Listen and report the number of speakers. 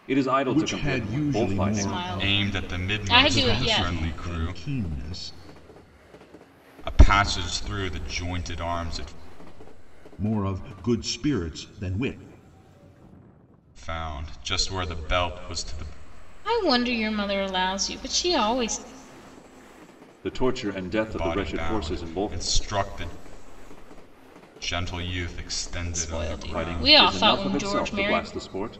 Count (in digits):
4